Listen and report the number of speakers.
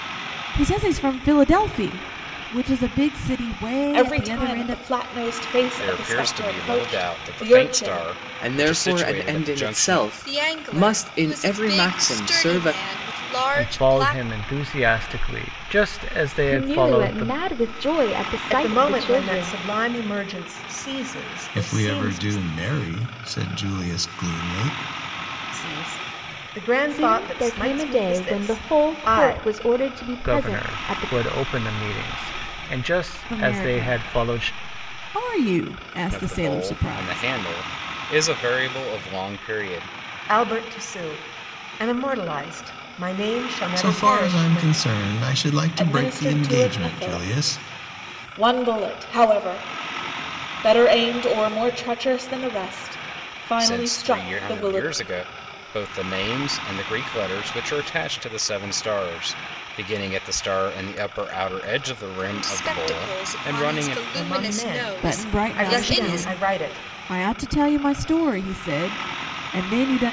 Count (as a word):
nine